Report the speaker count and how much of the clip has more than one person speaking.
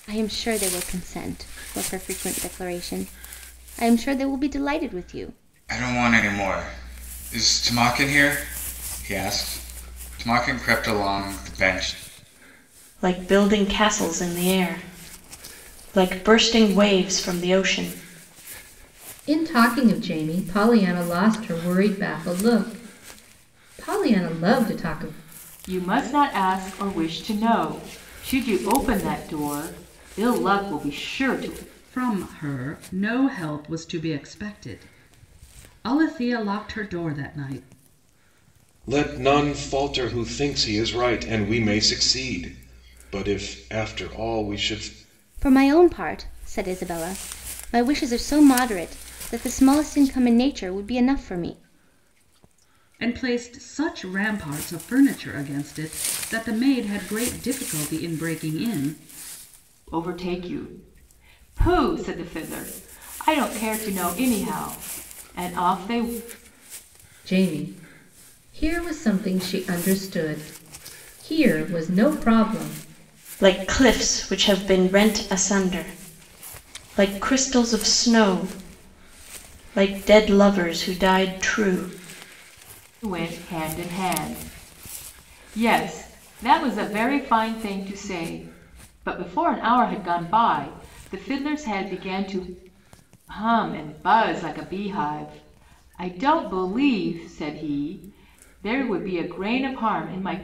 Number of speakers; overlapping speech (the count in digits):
7, no overlap